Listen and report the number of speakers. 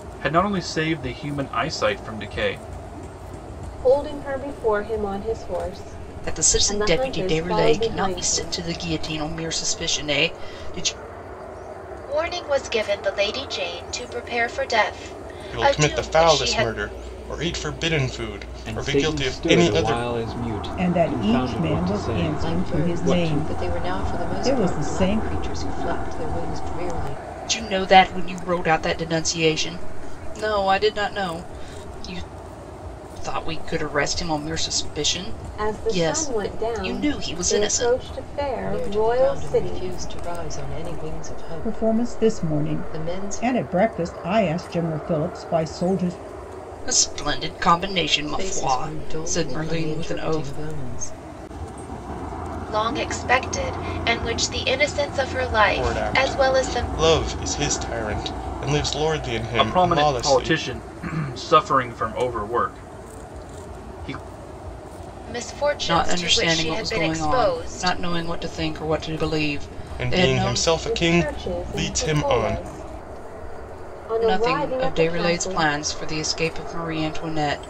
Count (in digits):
8